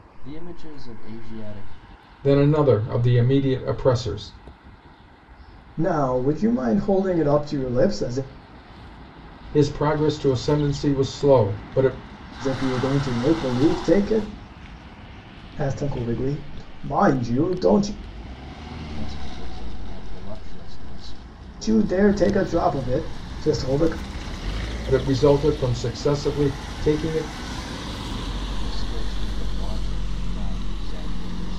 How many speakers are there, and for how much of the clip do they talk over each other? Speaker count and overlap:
3, no overlap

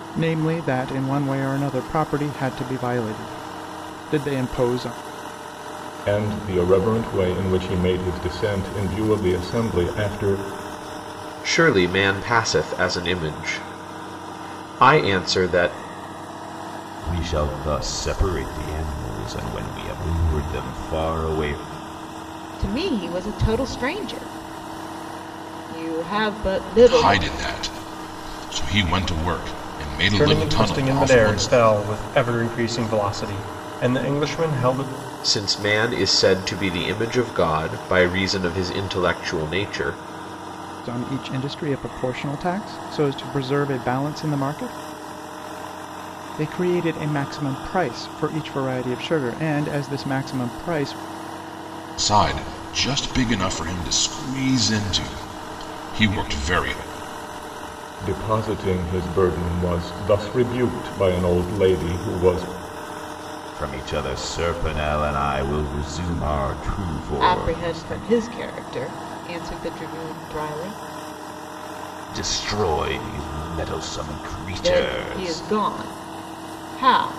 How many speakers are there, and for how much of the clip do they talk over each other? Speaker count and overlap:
7, about 5%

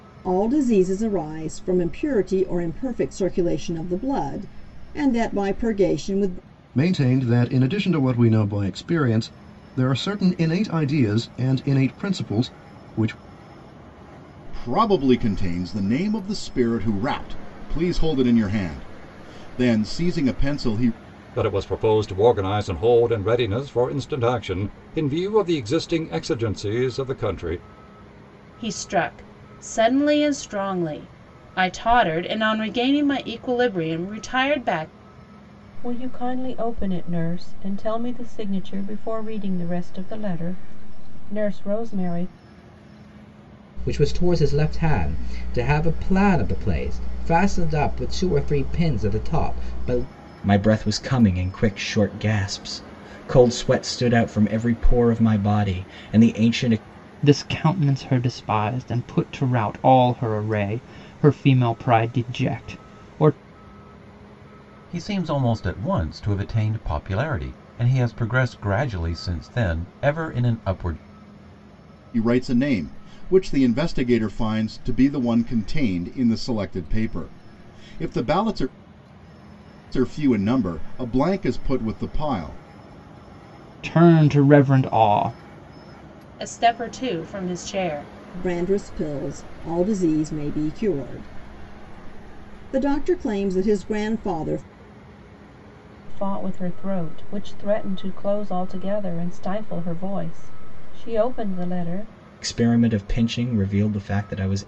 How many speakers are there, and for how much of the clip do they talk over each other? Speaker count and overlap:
10, no overlap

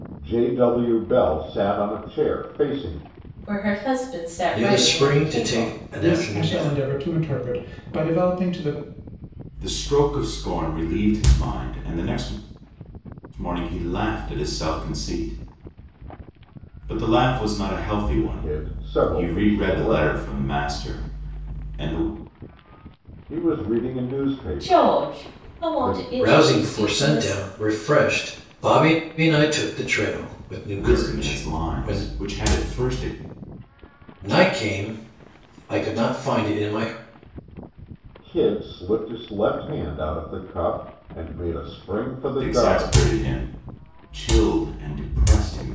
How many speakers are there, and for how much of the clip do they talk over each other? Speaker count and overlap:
5, about 20%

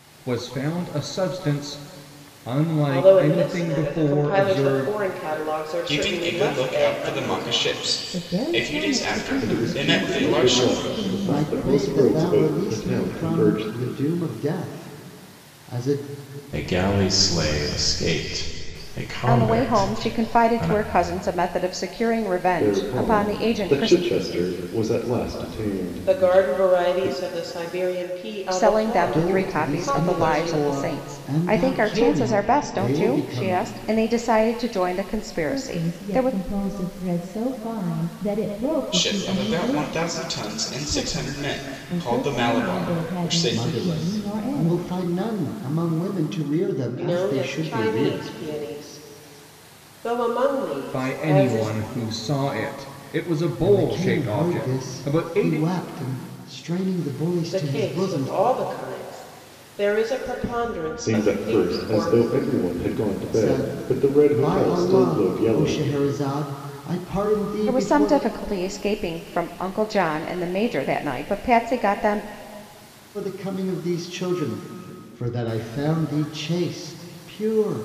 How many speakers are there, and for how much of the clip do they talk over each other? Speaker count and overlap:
8, about 44%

